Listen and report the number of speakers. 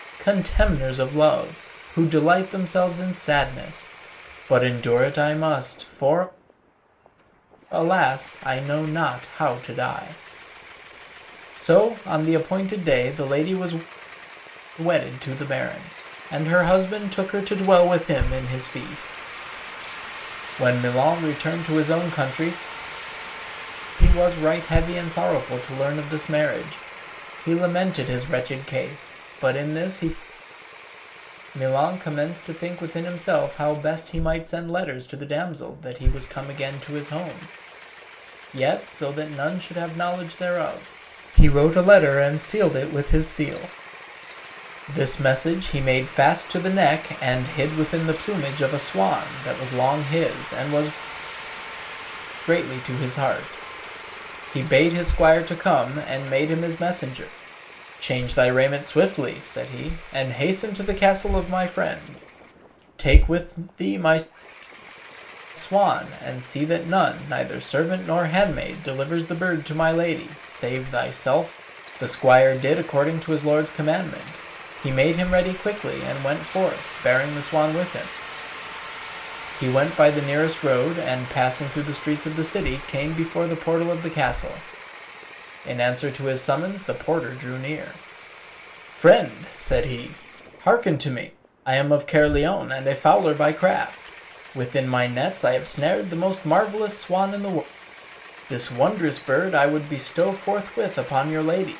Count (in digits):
1